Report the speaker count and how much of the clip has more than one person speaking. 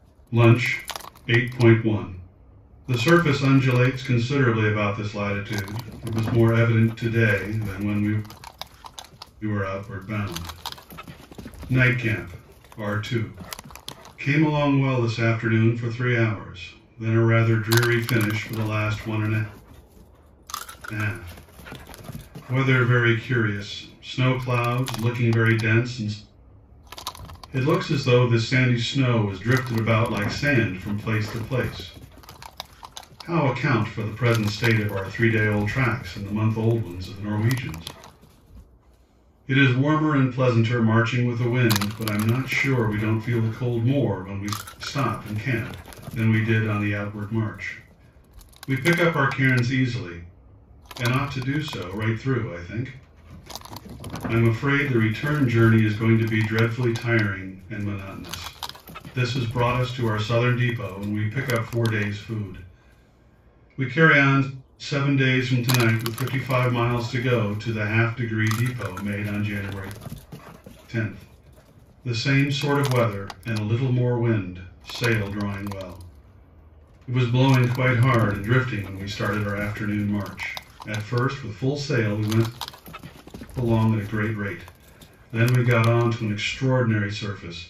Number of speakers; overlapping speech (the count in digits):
1, no overlap